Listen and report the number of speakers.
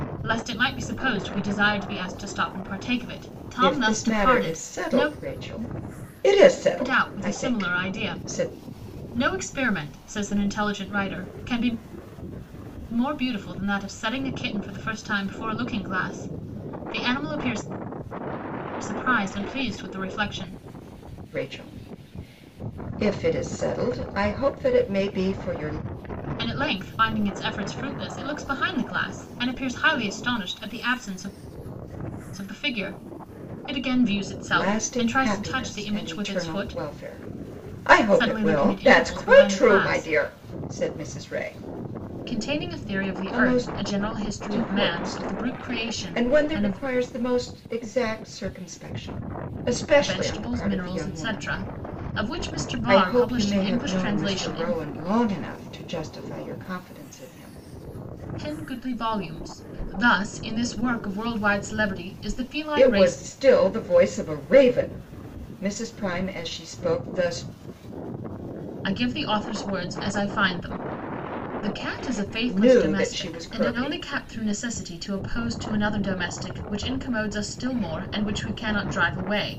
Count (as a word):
two